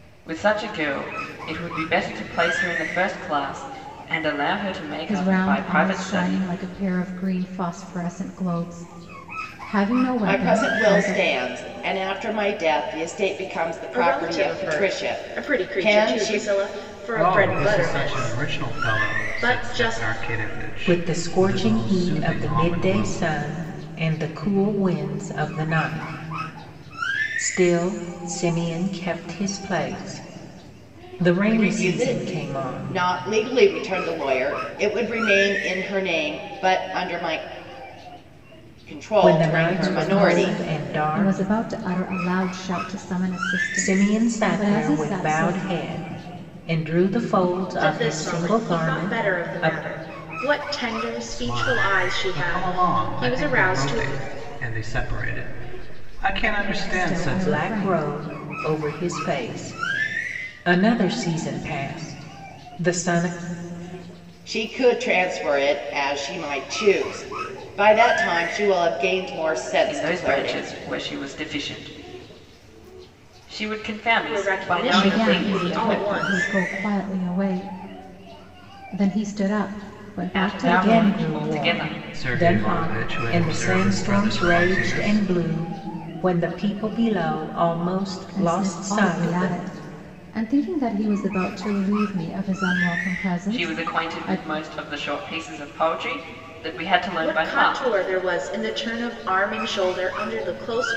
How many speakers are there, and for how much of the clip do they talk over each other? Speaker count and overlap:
6, about 32%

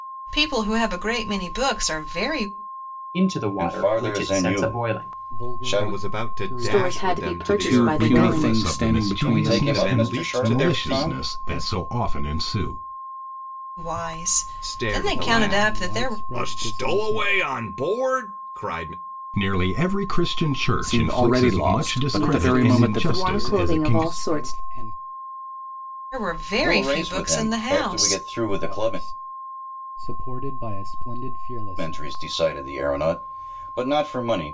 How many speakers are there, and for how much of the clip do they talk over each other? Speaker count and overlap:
8, about 50%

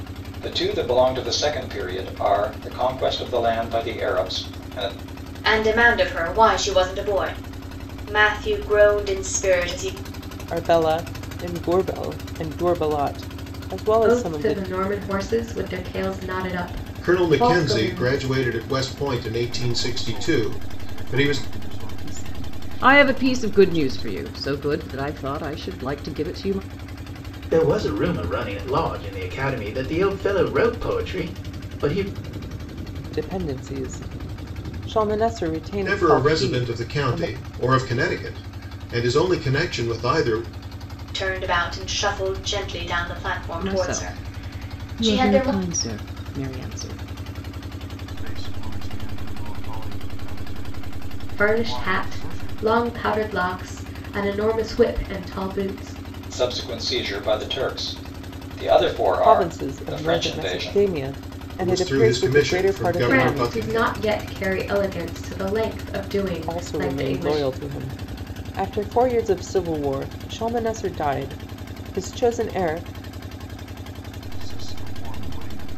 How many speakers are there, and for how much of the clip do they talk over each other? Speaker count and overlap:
8, about 21%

